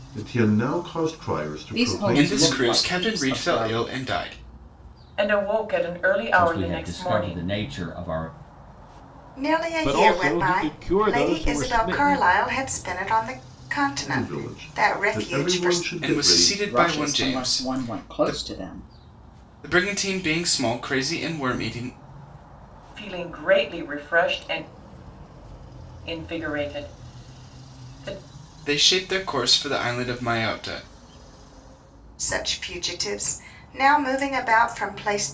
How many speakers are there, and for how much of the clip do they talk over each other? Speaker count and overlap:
seven, about 28%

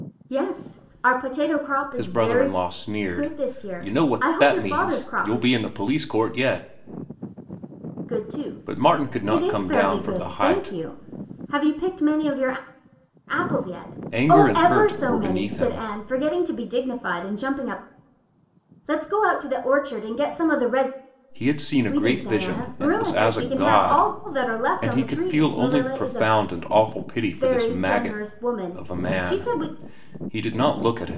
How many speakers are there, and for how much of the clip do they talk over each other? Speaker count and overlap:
two, about 43%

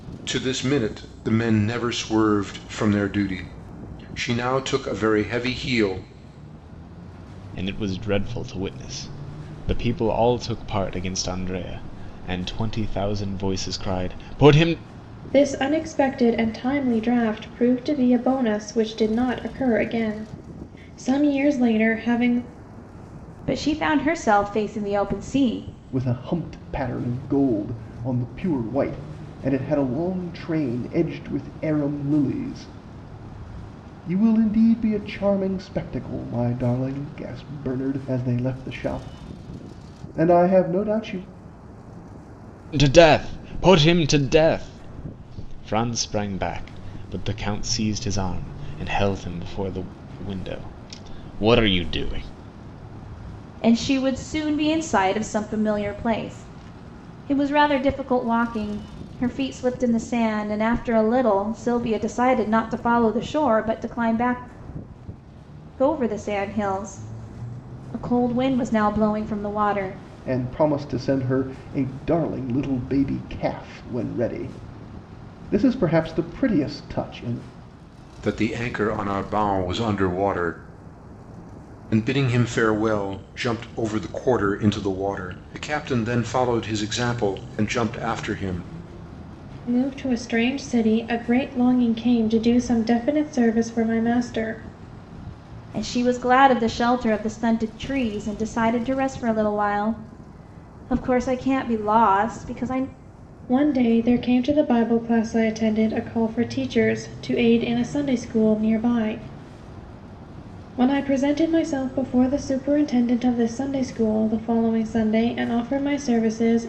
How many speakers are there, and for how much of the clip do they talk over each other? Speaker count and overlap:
five, no overlap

